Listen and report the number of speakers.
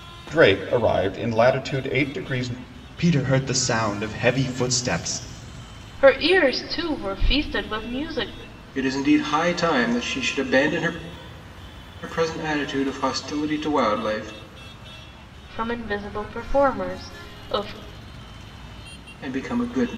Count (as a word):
four